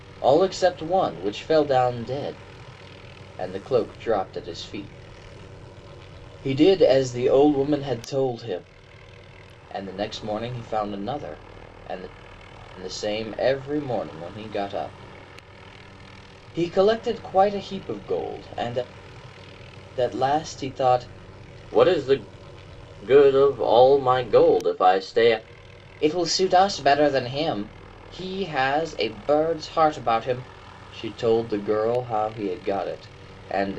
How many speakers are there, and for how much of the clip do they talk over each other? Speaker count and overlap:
1, no overlap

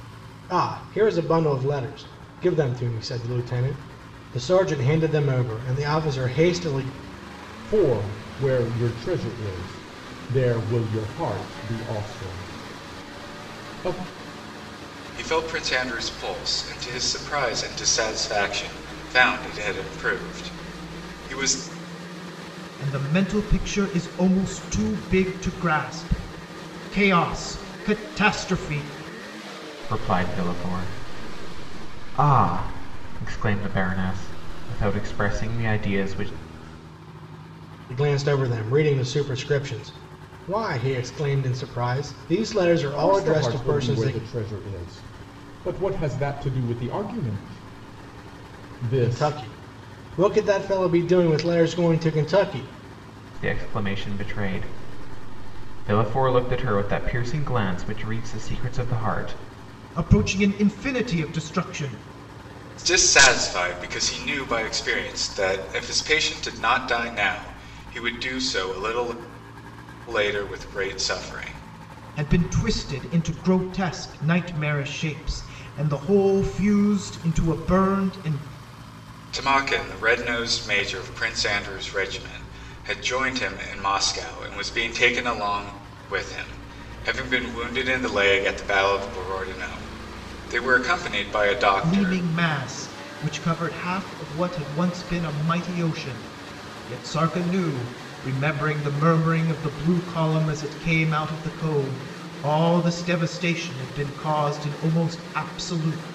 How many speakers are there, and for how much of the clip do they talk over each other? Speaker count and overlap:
5, about 2%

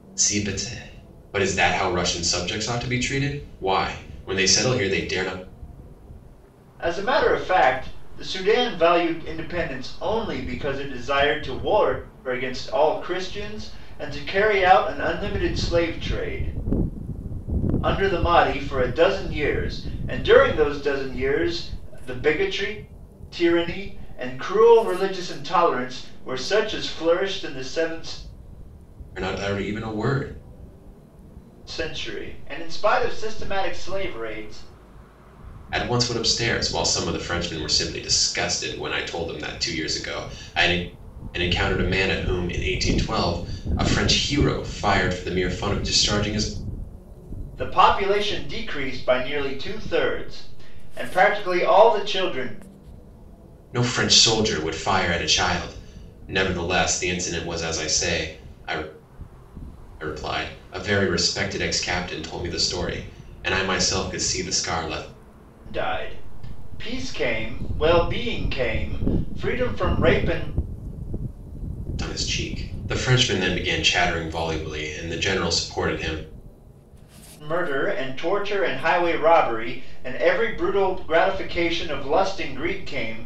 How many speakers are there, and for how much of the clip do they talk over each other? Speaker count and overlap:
2, no overlap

